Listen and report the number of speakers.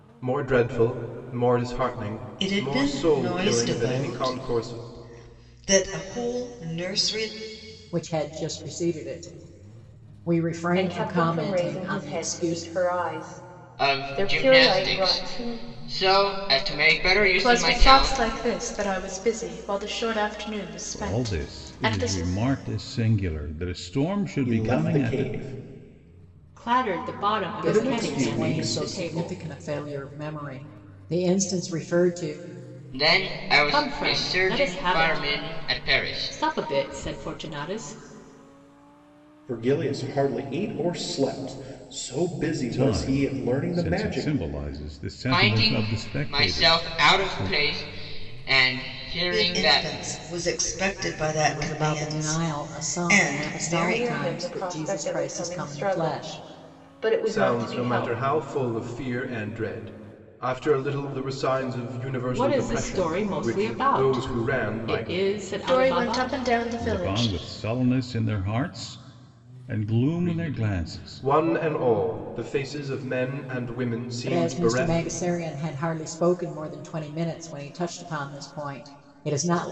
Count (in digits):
9